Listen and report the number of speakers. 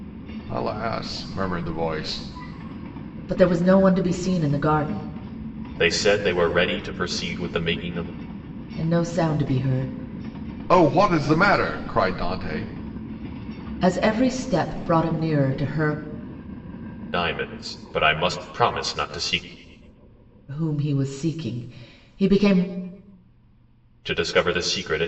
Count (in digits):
3